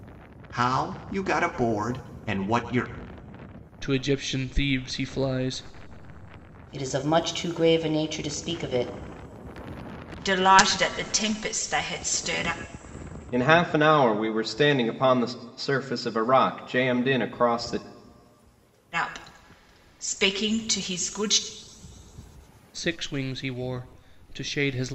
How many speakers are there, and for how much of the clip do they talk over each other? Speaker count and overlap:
five, no overlap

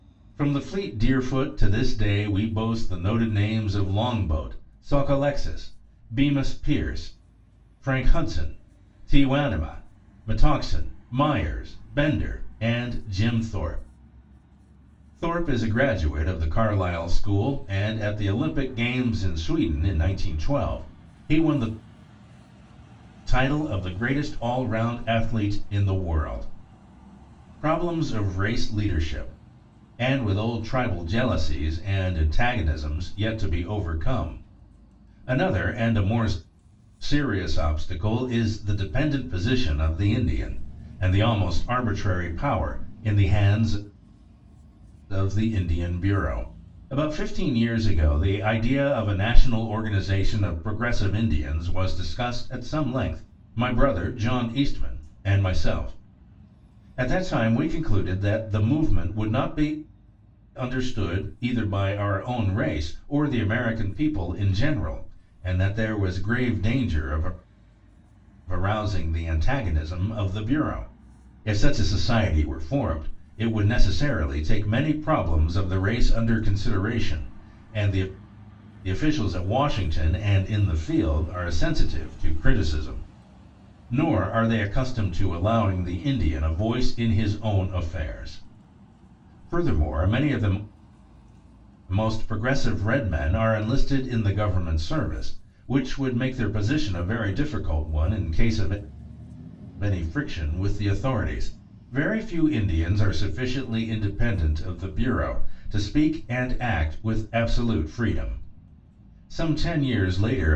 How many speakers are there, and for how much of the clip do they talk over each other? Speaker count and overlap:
one, no overlap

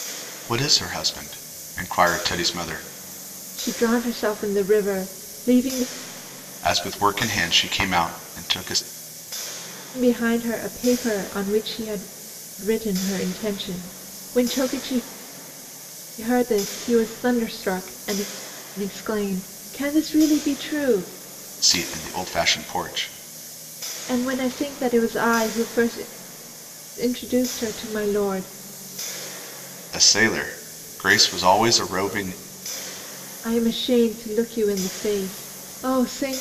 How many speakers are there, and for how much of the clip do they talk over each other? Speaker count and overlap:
two, no overlap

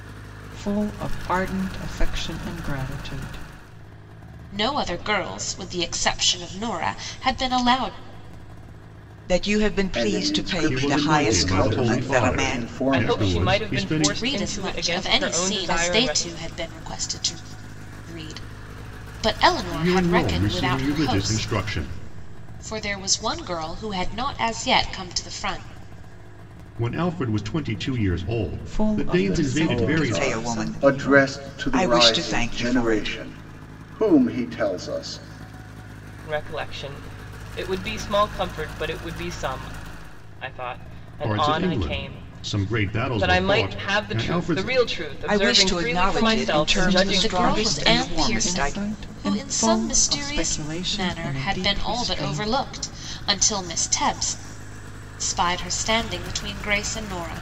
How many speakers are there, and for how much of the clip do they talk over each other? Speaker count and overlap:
six, about 40%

